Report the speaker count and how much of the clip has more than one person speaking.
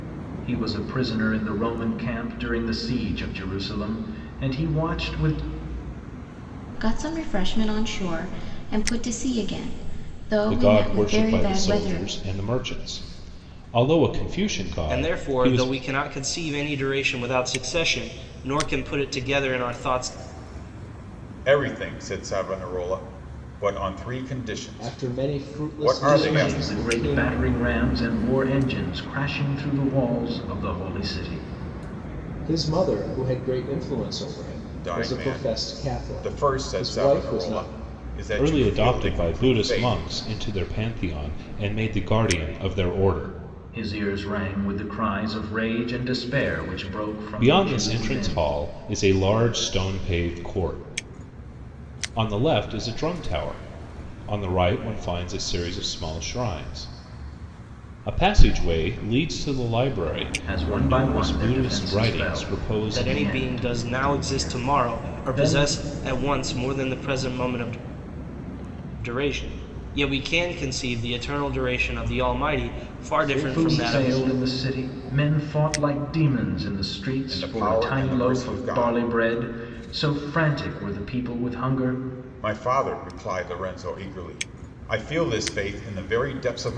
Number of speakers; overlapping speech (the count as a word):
six, about 22%